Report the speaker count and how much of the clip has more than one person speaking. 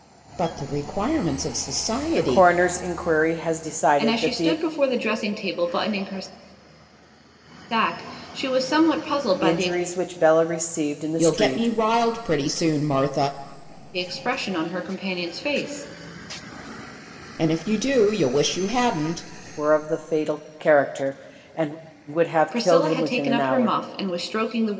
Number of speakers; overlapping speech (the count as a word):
three, about 13%